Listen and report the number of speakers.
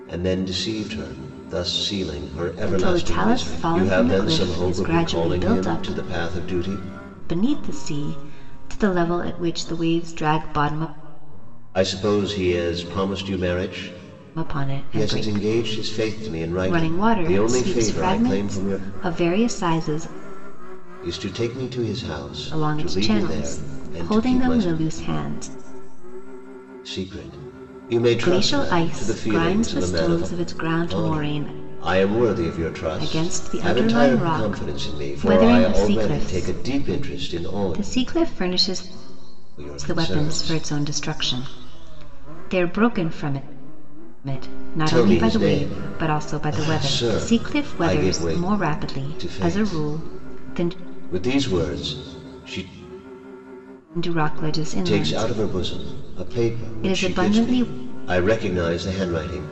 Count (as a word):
two